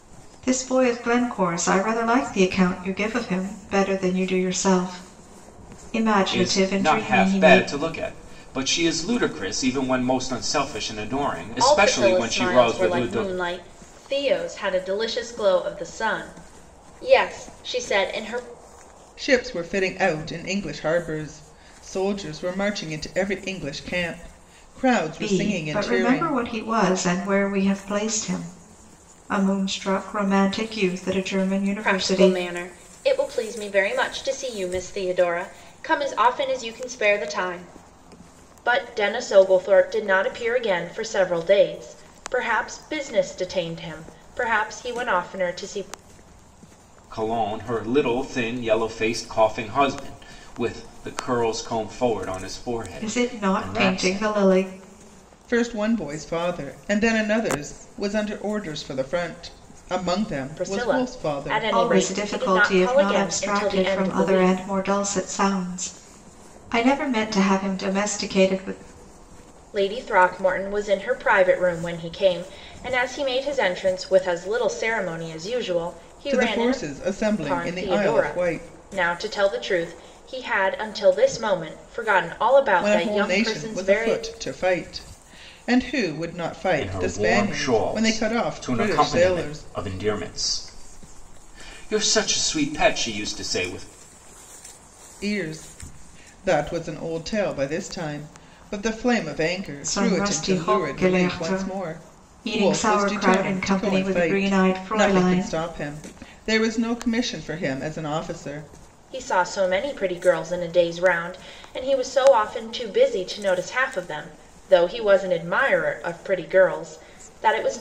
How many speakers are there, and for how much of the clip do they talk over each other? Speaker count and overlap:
4, about 19%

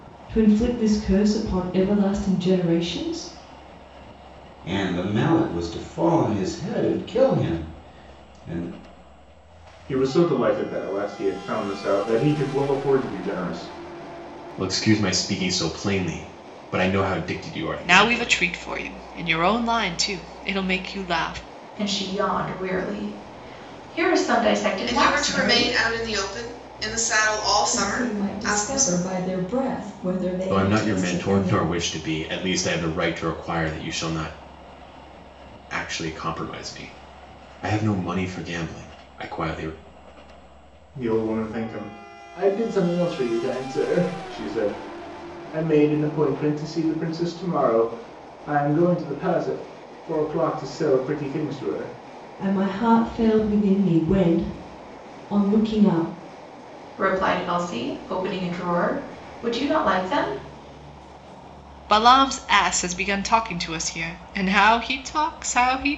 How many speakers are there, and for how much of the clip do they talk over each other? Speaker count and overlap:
8, about 6%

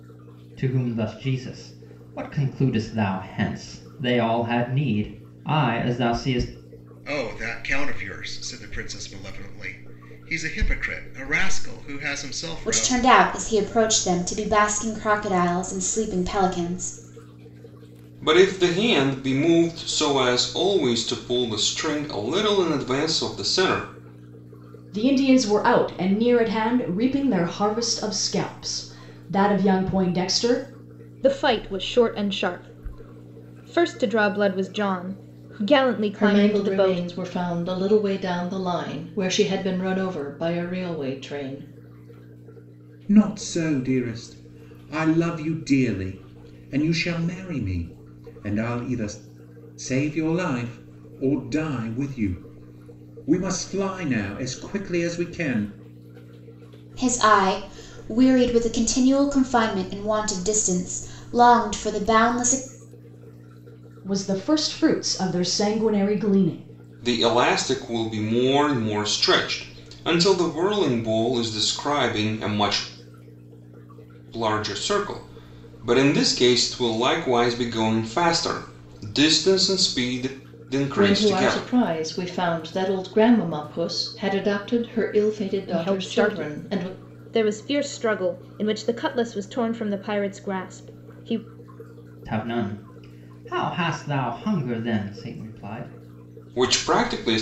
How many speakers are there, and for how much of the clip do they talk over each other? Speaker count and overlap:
8, about 4%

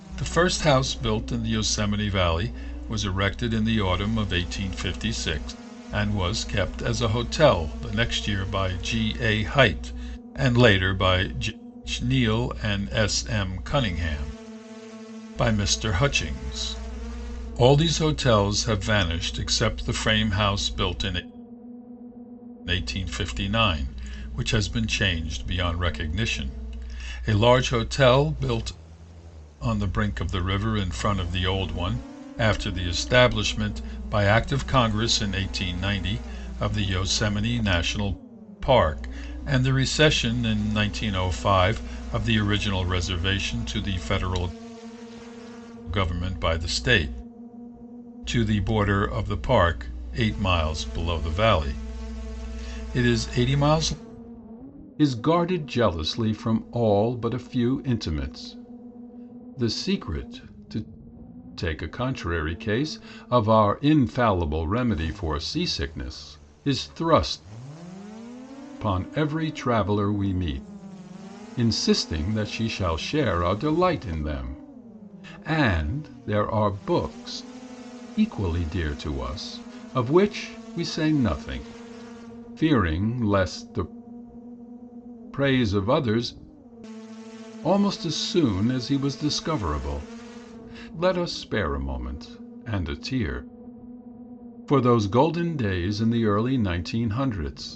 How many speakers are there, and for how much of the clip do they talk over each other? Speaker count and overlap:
1, no overlap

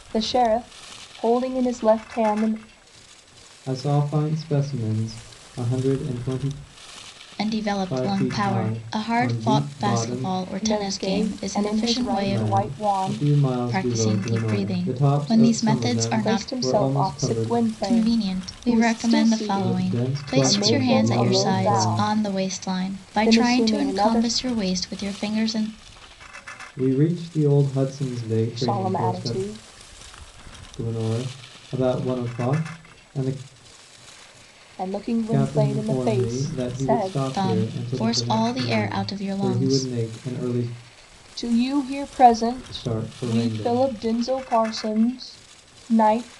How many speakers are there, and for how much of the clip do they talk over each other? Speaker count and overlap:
3, about 48%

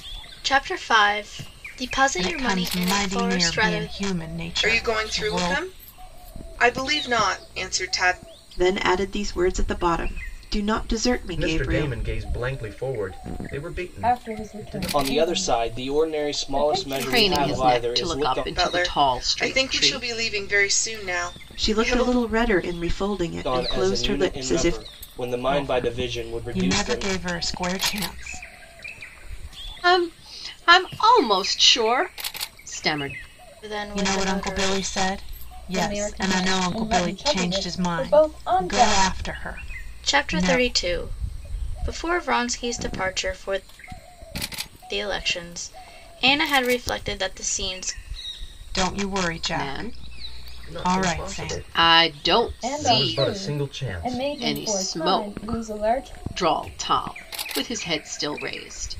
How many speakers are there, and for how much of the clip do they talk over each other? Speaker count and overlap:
8, about 42%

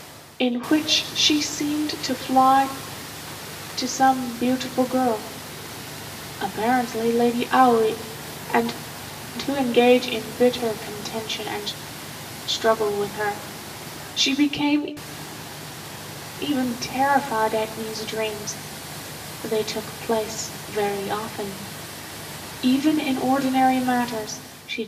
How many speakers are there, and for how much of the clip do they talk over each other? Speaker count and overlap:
1, no overlap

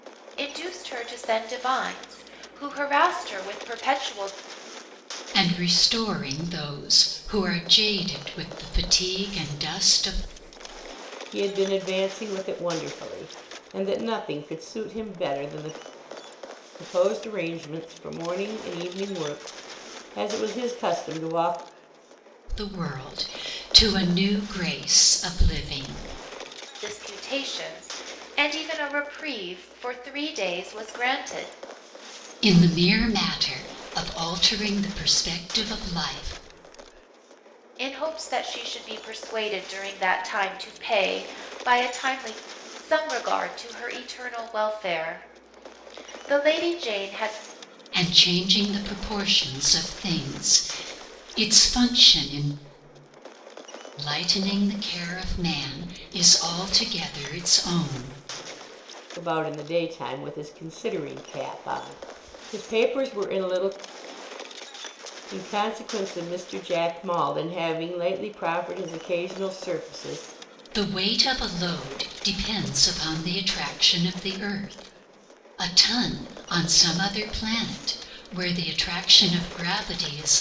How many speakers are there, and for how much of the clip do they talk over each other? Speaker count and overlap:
3, no overlap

